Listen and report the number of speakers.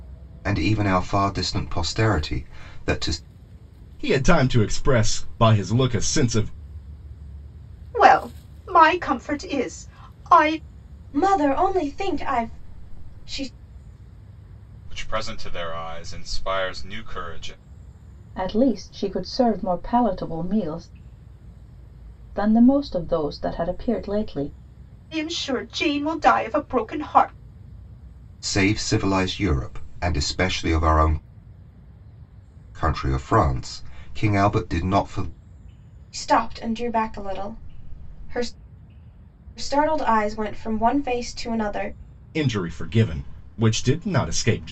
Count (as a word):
six